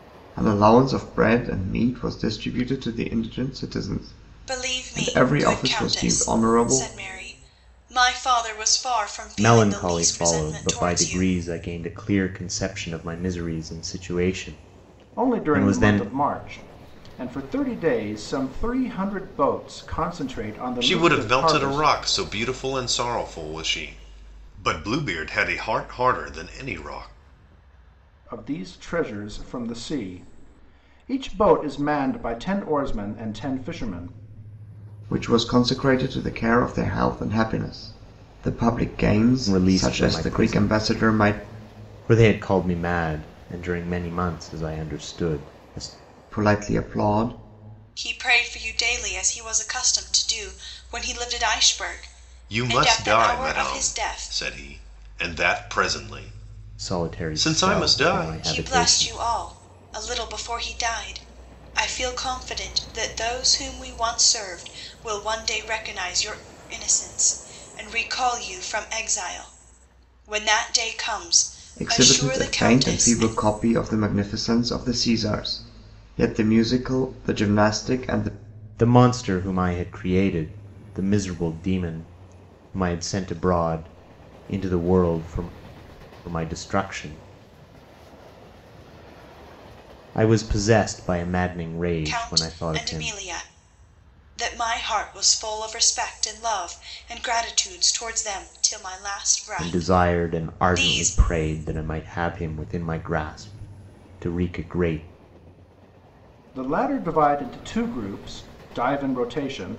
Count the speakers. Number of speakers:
5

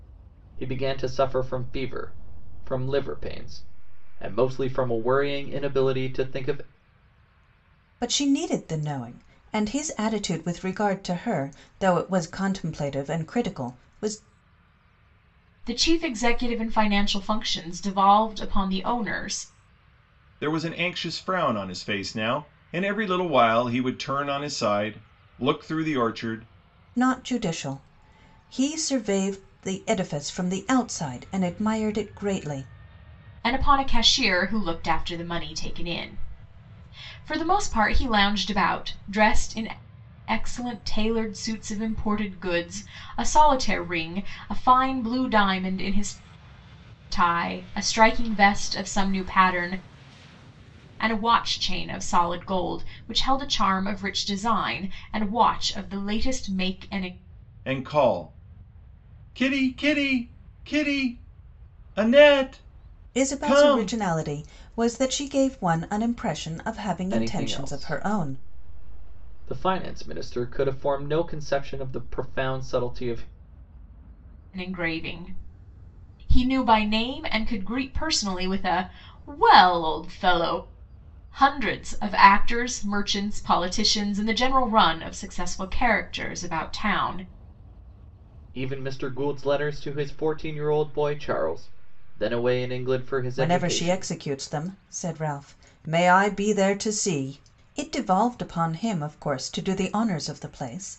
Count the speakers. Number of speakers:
4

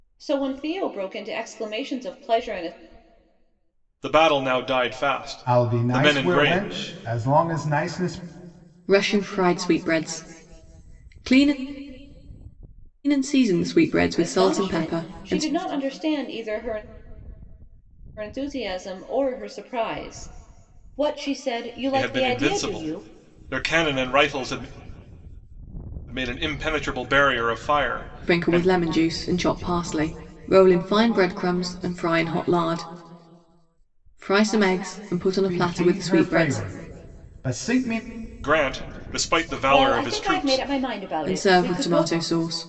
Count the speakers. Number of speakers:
4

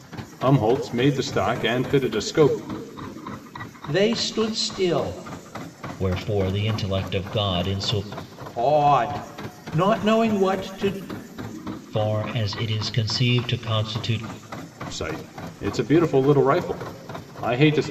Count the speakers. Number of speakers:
3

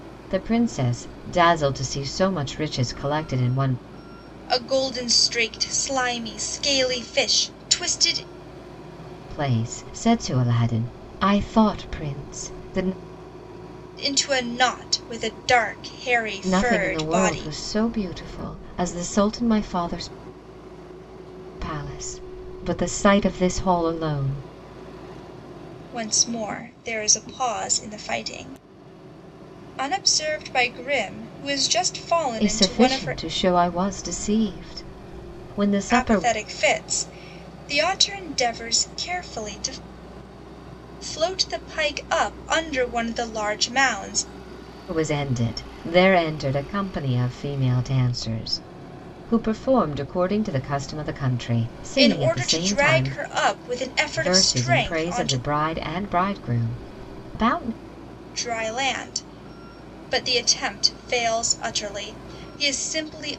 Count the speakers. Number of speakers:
2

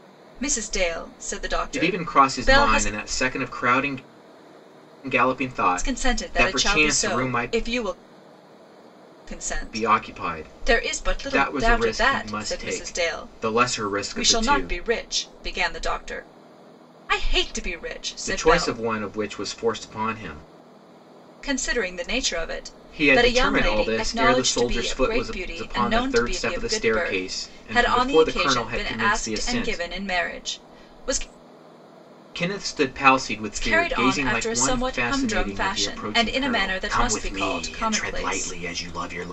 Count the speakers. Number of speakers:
2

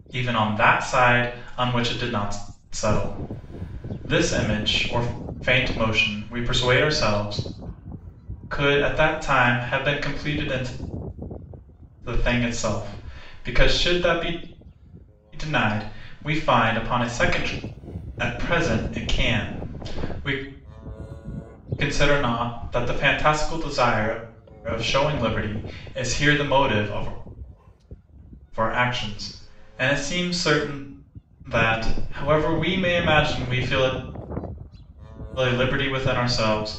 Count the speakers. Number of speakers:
1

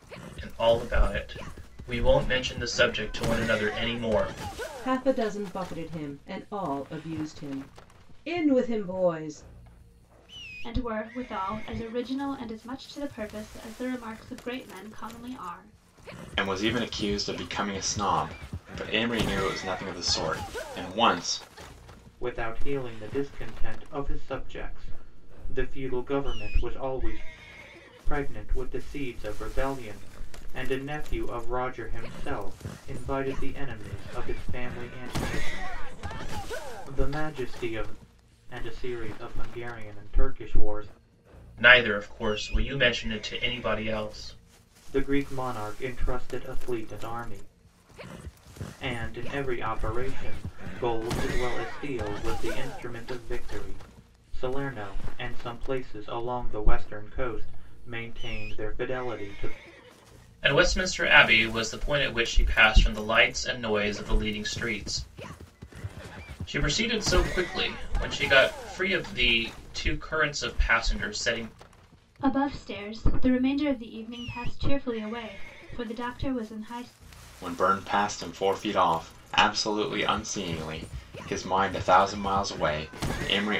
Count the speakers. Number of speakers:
5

